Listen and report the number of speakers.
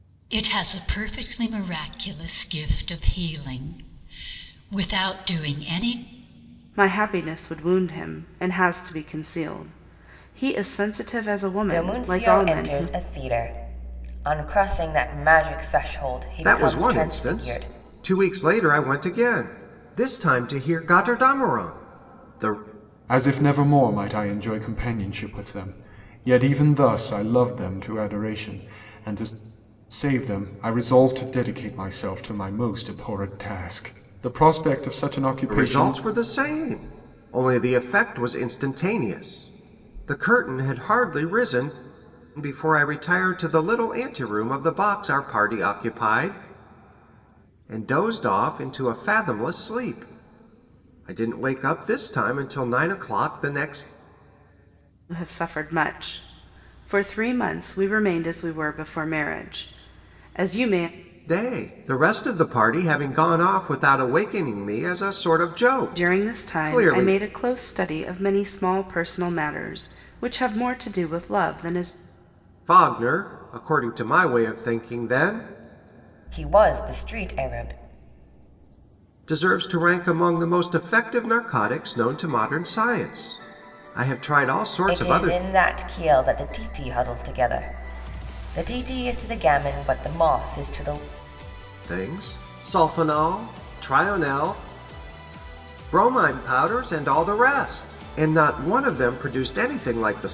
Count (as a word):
five